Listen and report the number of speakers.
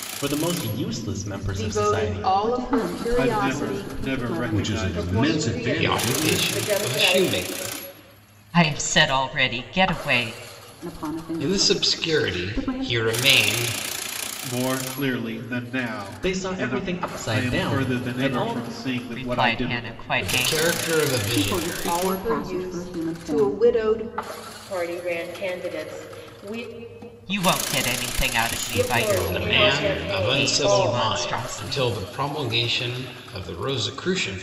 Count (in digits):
8